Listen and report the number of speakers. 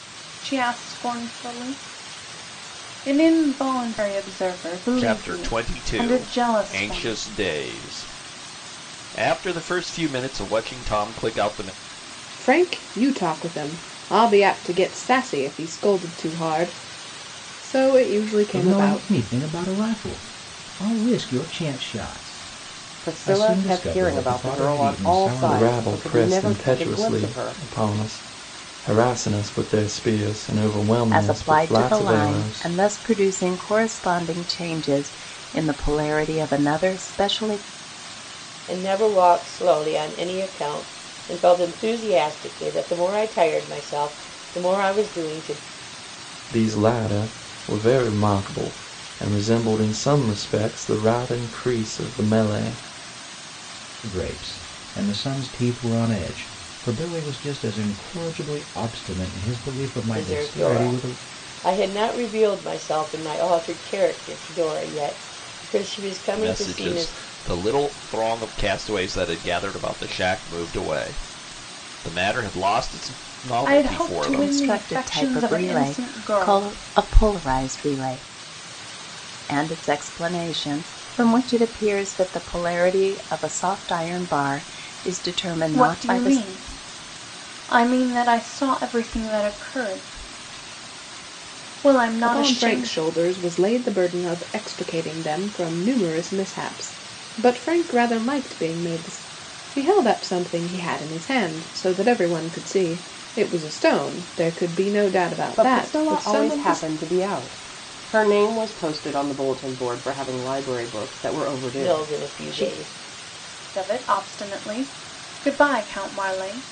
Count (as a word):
eight